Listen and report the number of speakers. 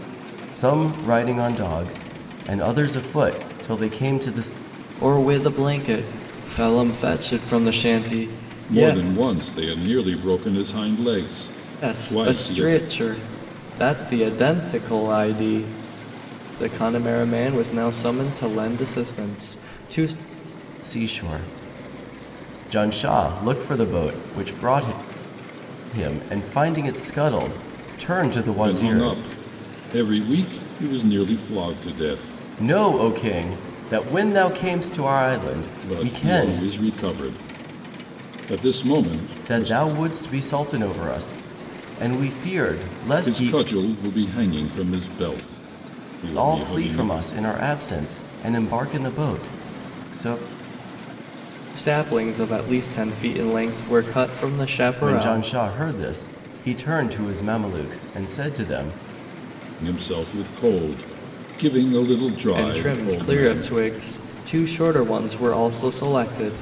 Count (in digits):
3